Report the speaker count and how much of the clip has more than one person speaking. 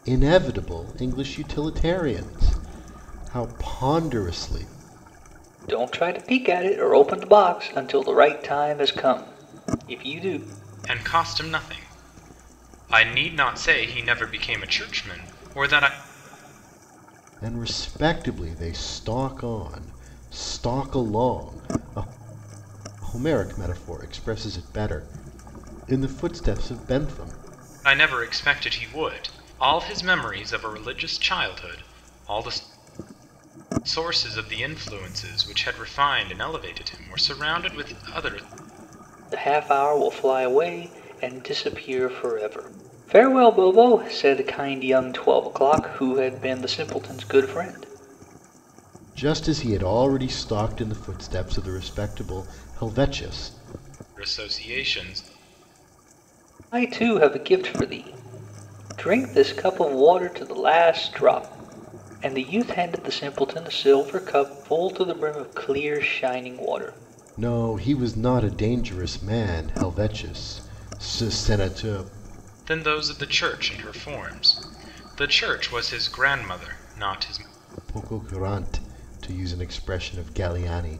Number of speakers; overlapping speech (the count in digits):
3, no overlap